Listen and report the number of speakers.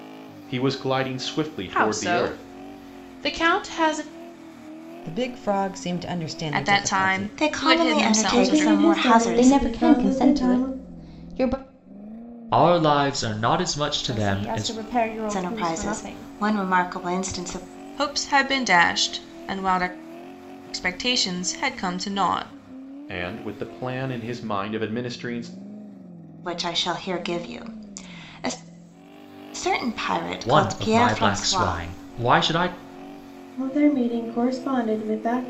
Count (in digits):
9